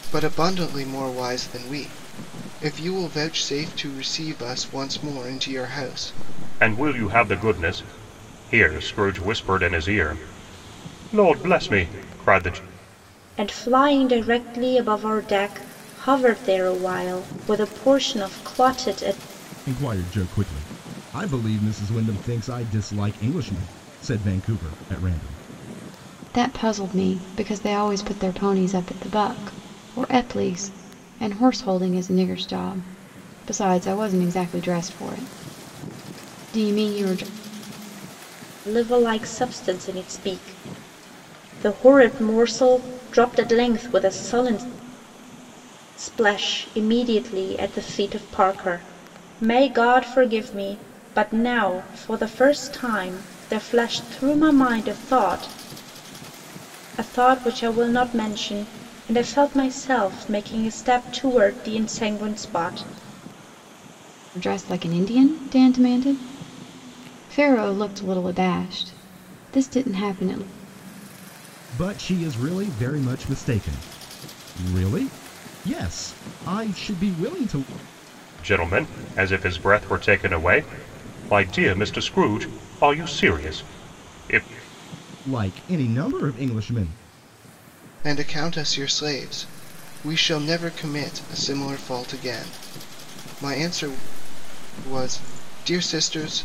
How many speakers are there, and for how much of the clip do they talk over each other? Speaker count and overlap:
five, no overlap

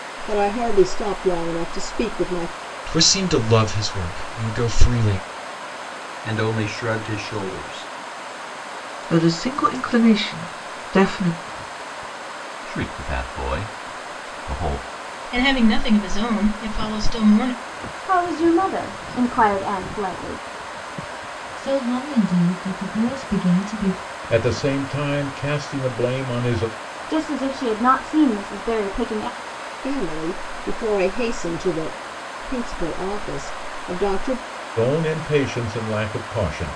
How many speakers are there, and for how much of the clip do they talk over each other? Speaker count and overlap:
nine, no overlap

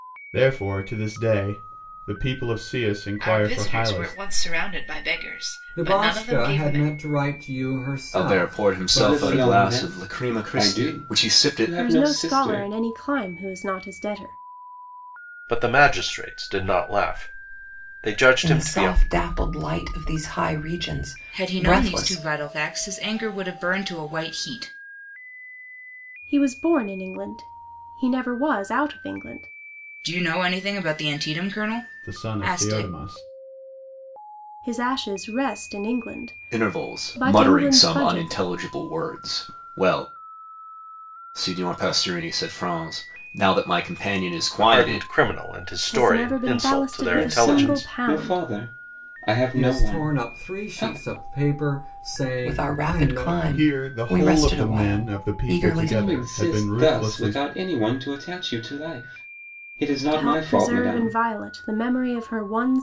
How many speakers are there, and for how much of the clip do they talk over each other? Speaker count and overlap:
nine, about 35%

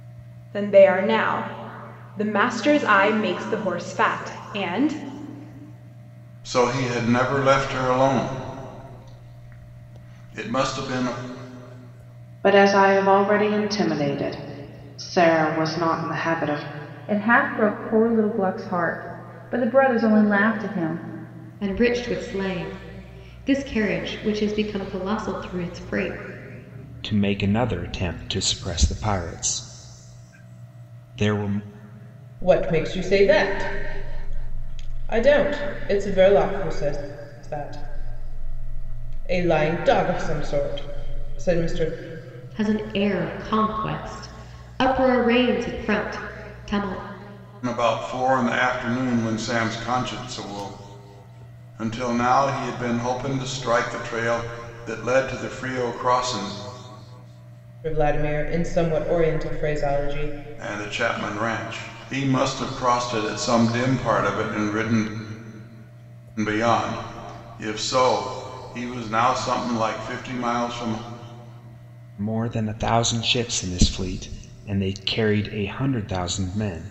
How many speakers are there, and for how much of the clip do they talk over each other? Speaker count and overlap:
seven, no overlap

